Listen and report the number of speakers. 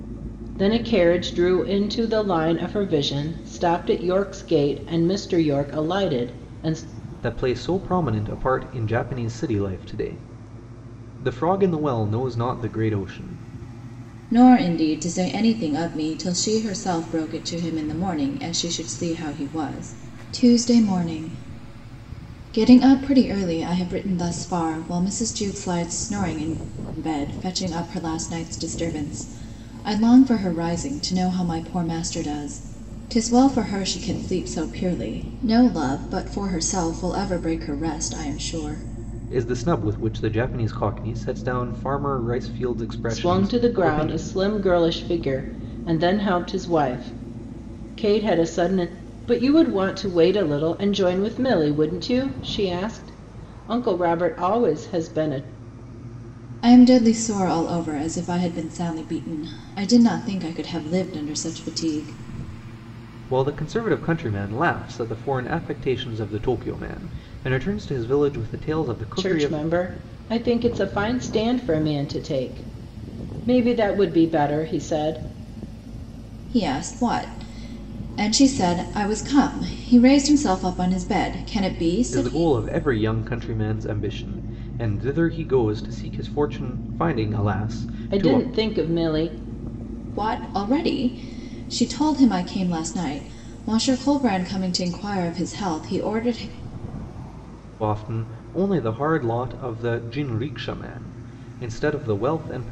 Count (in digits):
3